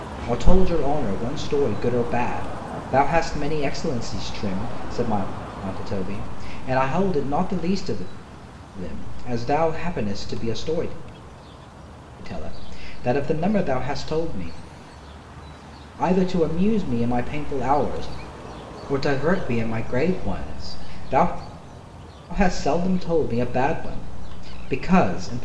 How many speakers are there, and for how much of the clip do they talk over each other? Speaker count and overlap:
one, no overlap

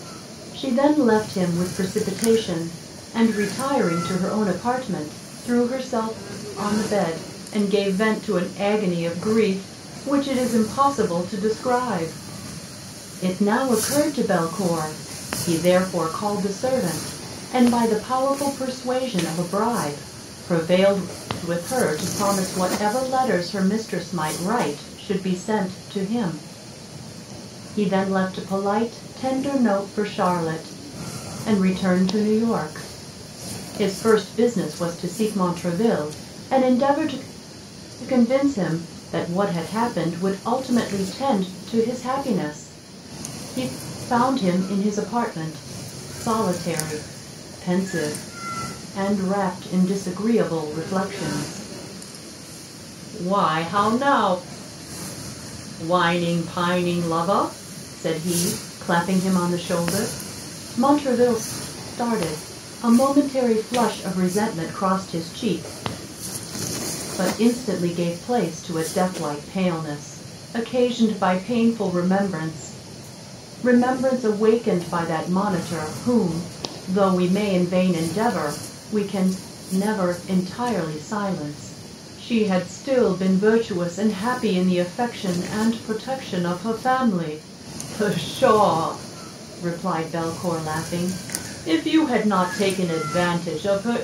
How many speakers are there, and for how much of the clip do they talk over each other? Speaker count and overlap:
one, no overlap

